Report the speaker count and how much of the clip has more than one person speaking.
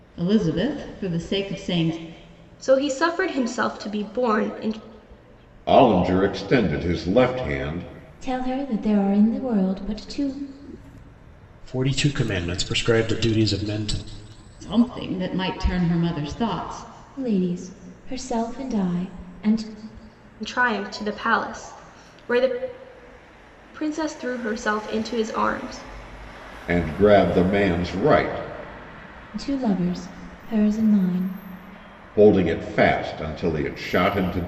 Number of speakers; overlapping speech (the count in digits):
5, no overlap